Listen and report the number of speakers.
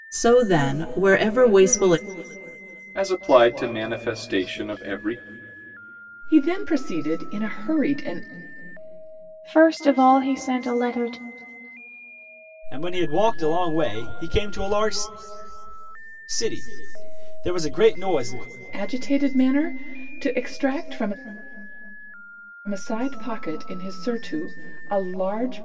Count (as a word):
five